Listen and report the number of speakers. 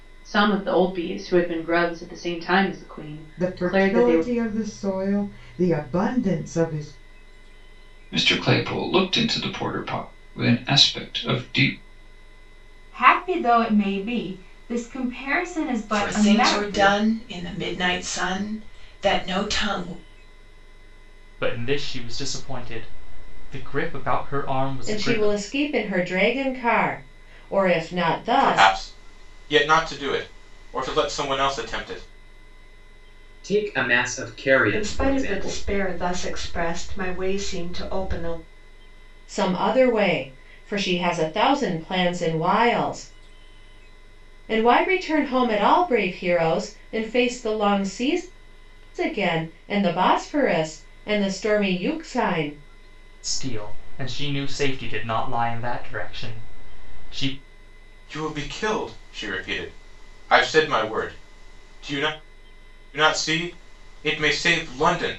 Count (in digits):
10